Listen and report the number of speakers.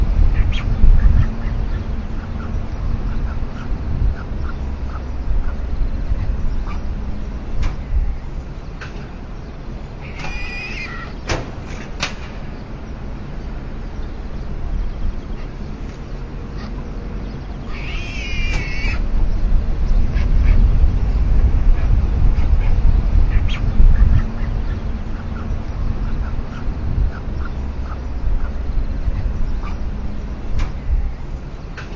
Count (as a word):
zero